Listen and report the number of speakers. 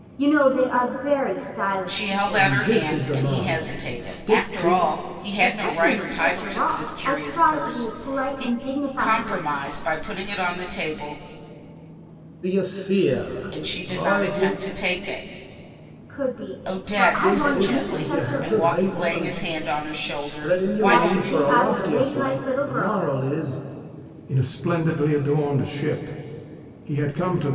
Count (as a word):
three